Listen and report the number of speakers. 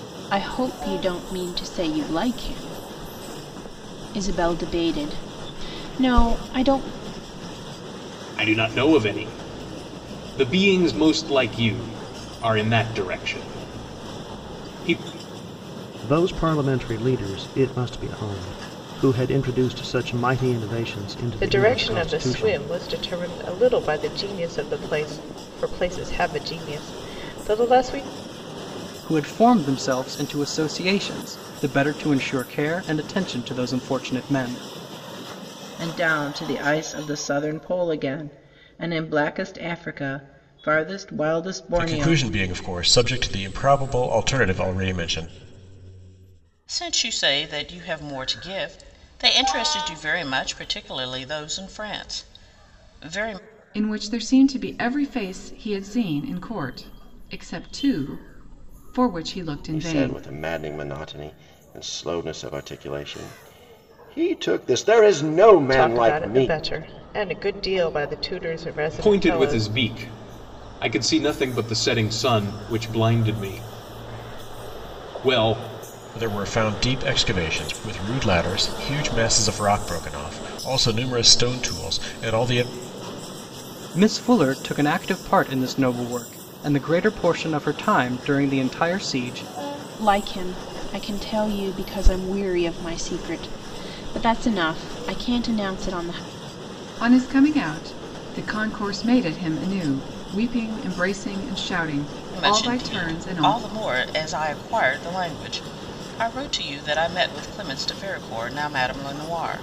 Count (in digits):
10